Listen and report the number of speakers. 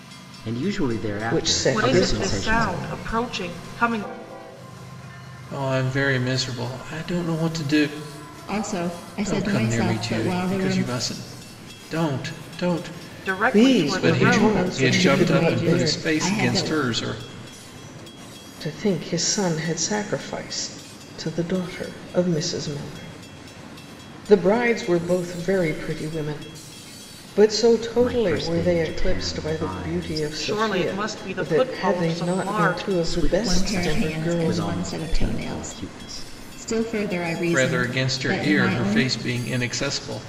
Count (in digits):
5